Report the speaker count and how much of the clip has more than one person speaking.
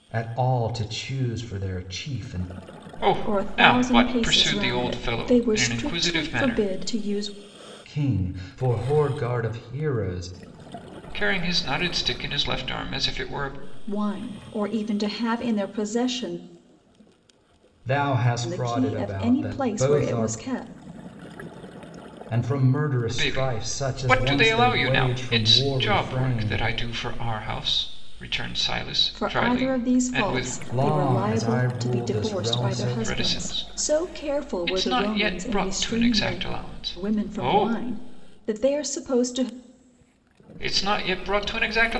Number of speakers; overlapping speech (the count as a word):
three, about 39%